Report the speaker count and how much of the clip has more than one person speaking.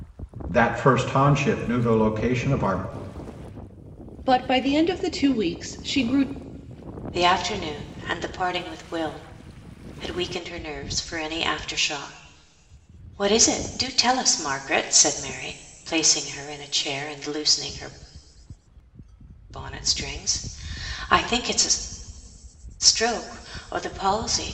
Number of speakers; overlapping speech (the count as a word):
three, no overlap